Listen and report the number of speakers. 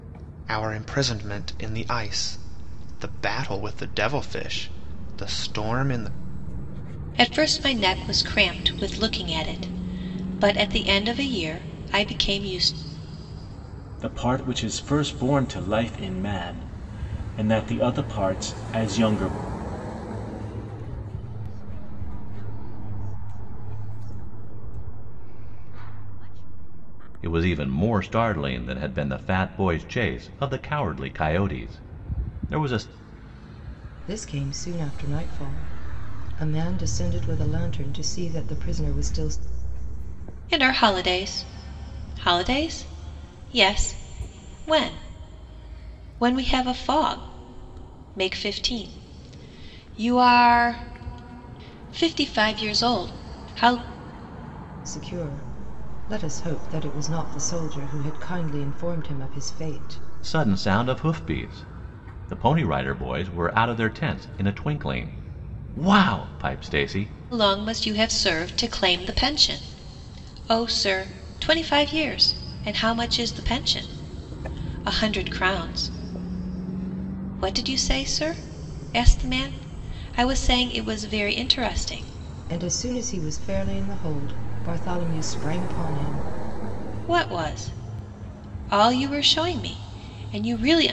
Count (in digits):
6